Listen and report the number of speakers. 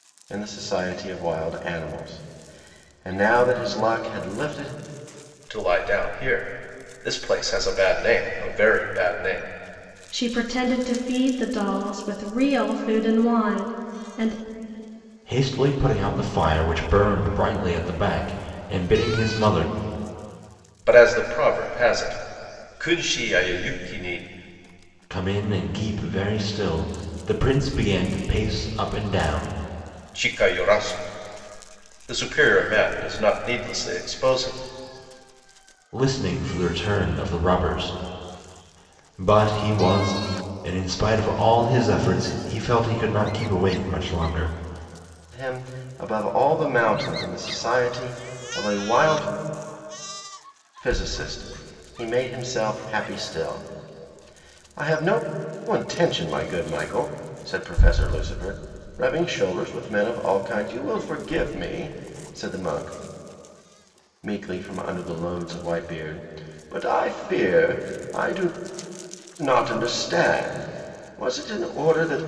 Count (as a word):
four